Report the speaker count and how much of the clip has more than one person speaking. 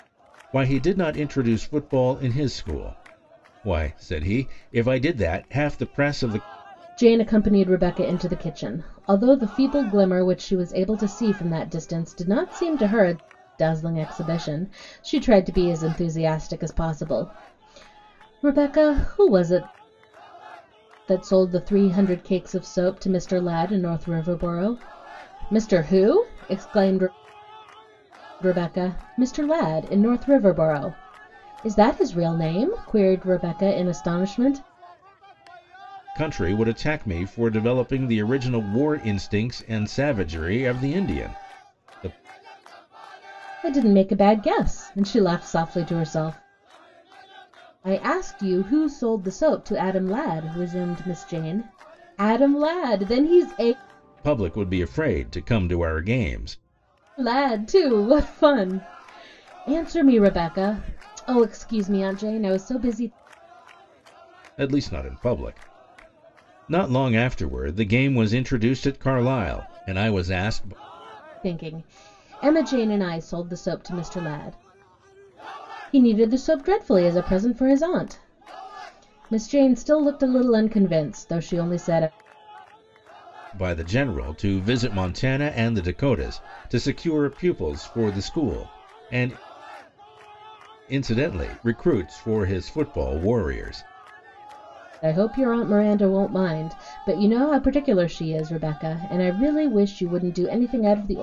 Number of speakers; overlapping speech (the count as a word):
two, no overlap